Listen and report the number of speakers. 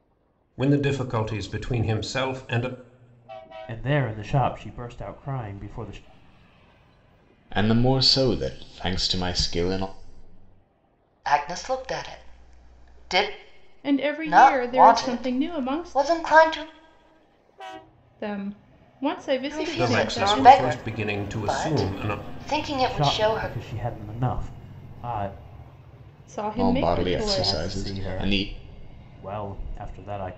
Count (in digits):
5